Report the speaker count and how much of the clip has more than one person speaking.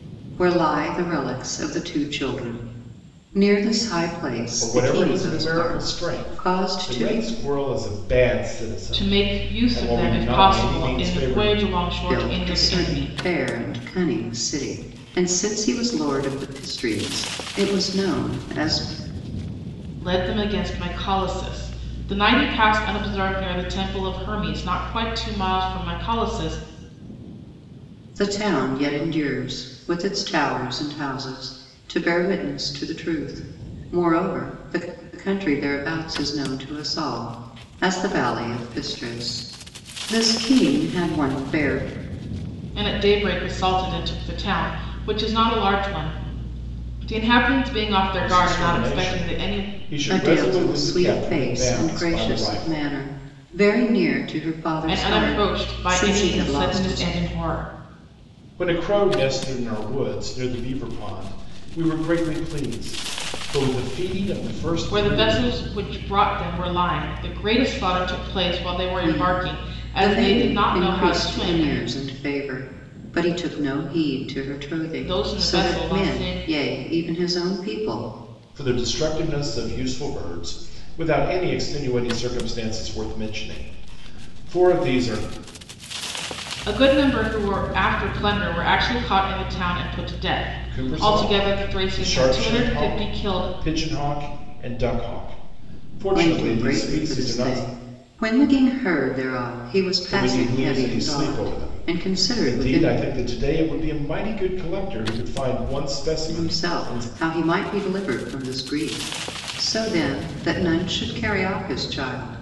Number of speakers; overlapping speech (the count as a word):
three, about 23%